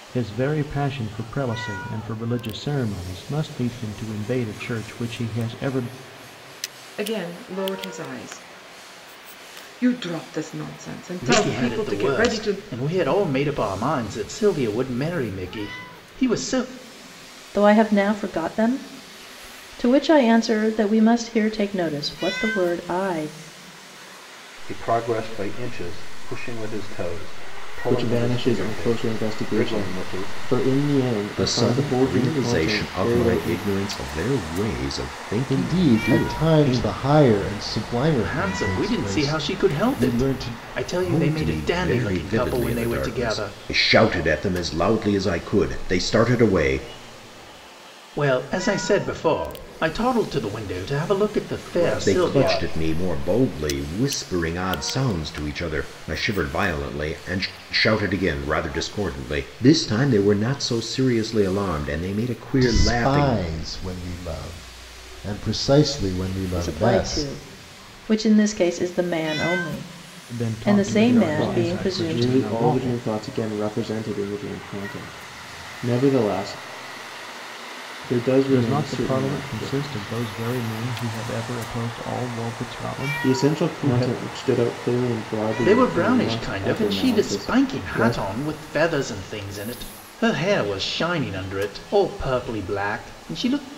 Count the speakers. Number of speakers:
eight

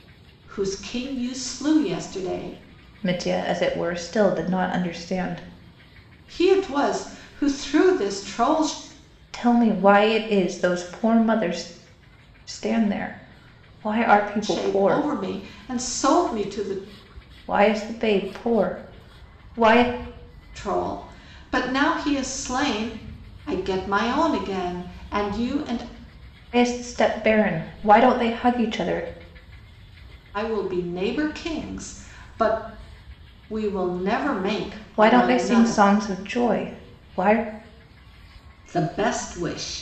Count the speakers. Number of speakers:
two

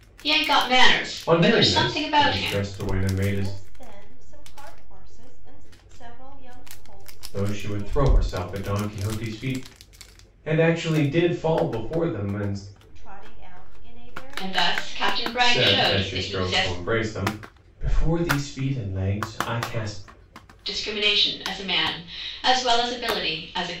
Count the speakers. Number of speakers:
three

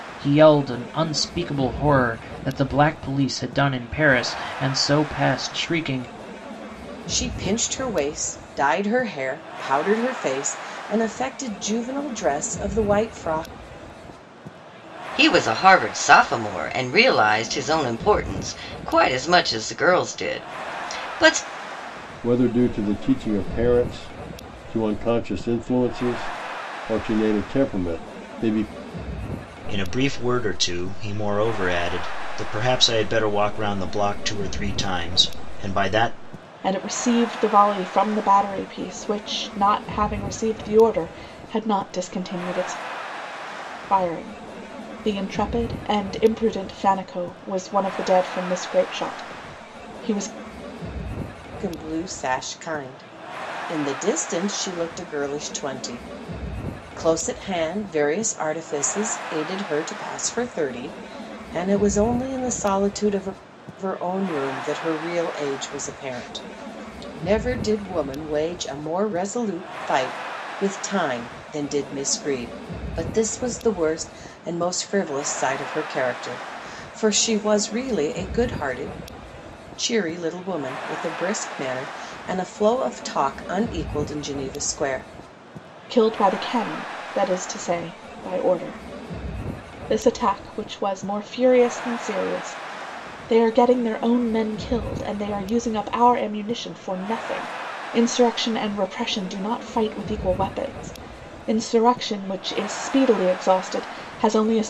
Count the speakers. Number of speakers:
six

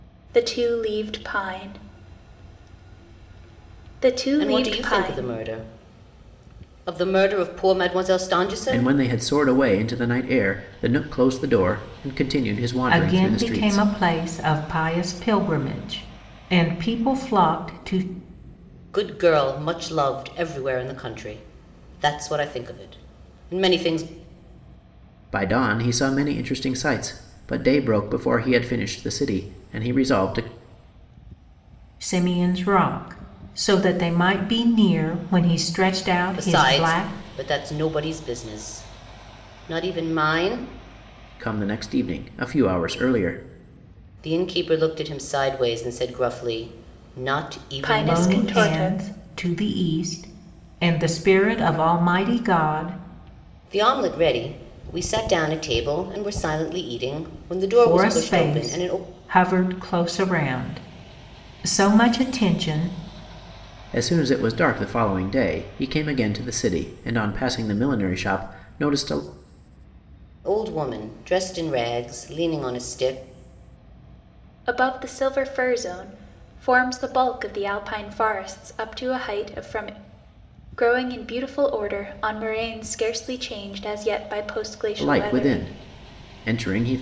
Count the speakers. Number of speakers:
four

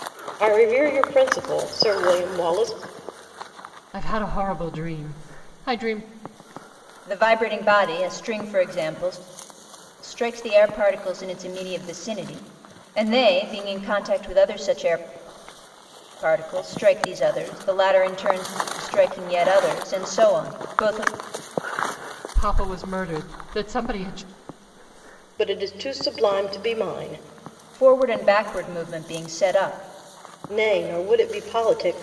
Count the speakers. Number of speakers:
three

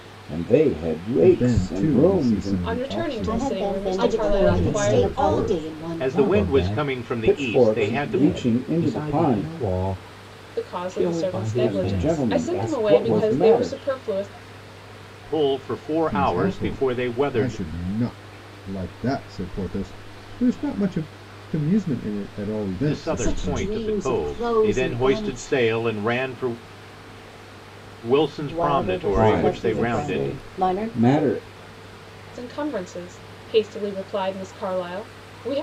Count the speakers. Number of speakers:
seven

